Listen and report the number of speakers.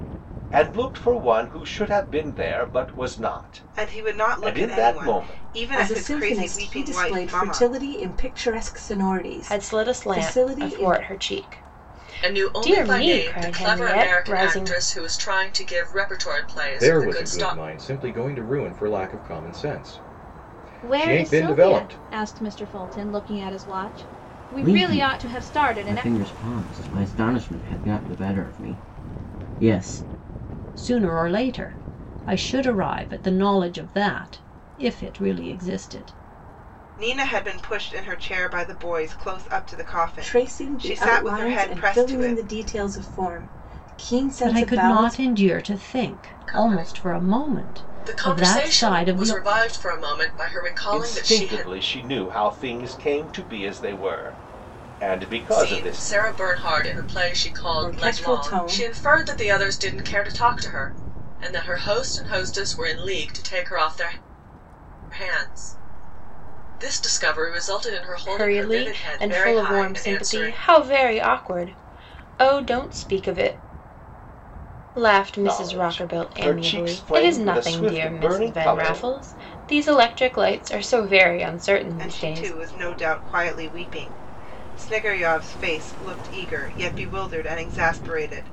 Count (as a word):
nine